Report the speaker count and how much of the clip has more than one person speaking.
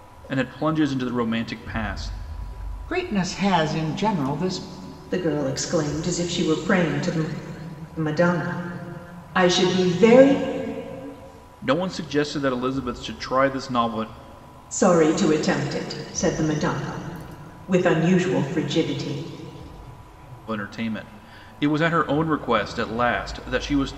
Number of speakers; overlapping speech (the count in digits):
3, no overlap